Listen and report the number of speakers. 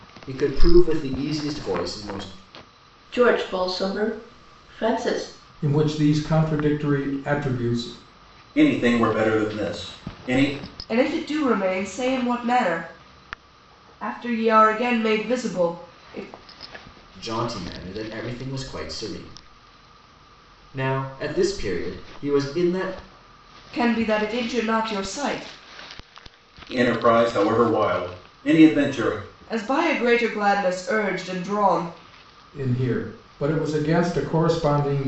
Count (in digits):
5